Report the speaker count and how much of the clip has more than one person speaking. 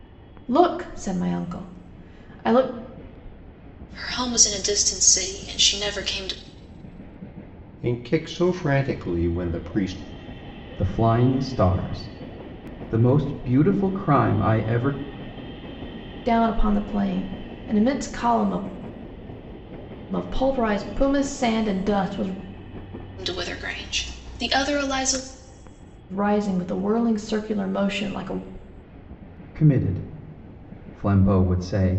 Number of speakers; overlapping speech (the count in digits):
4, no overlap